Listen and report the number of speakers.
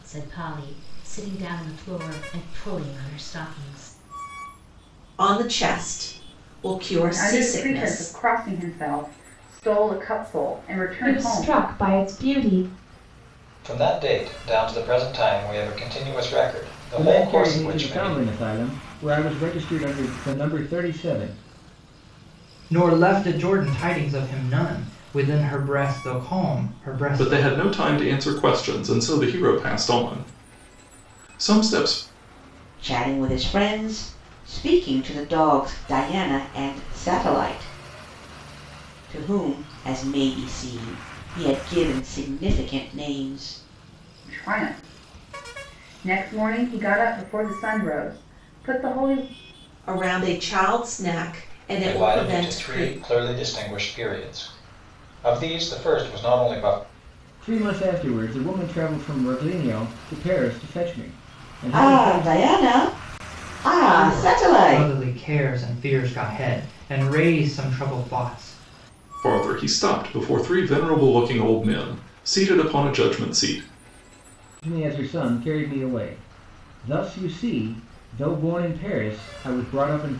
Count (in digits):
9